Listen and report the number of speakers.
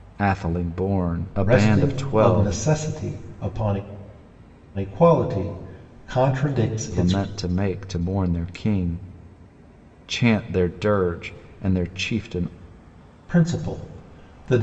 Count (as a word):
two